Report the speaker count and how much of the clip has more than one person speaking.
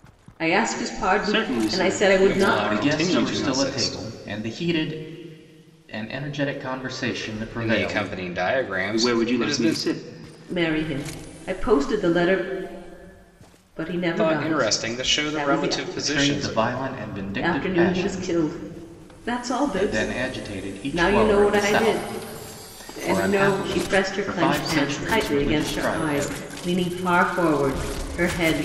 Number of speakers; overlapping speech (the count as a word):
four, about 47%